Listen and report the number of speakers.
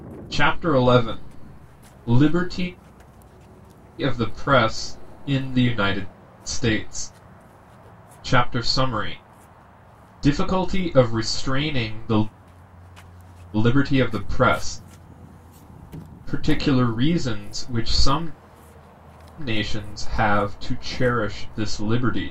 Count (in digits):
1